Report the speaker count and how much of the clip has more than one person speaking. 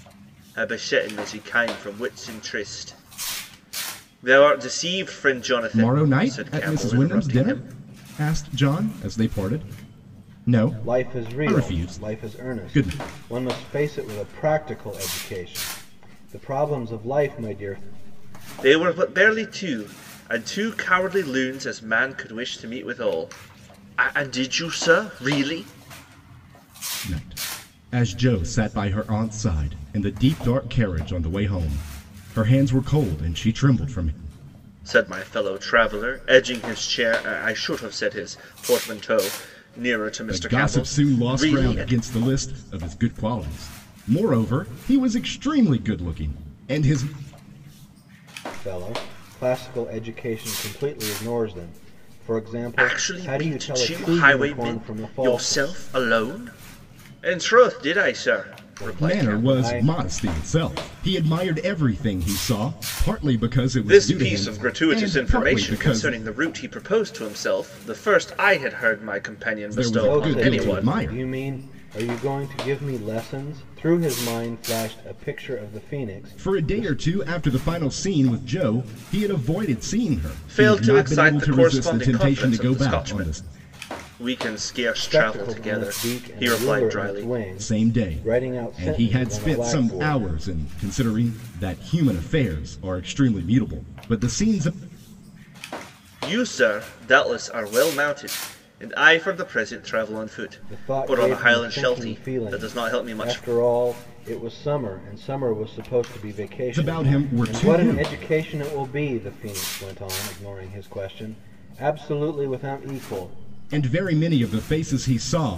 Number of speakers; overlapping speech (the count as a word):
three, about 23%